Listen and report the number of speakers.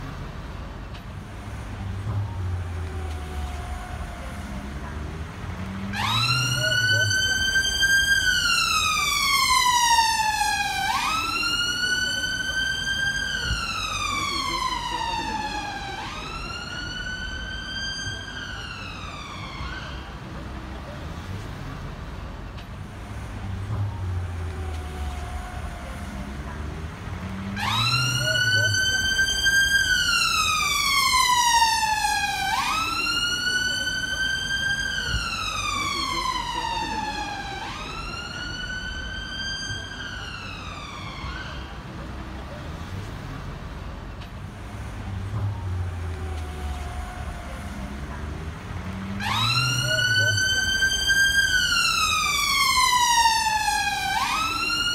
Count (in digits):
0